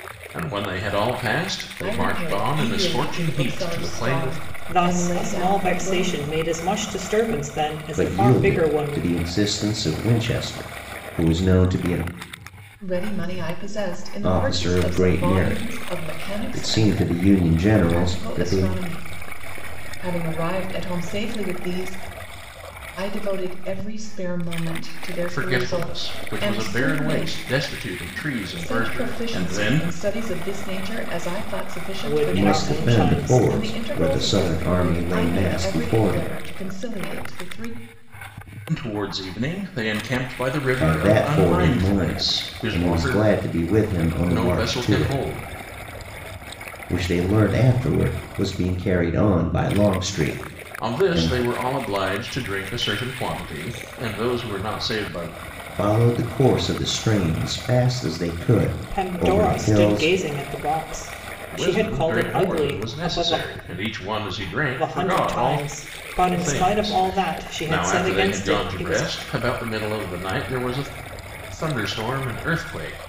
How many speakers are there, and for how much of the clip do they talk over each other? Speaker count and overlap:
4, about 38%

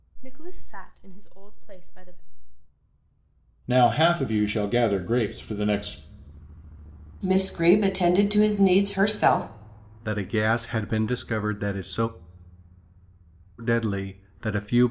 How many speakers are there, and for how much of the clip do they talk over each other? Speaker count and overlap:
4, no overlap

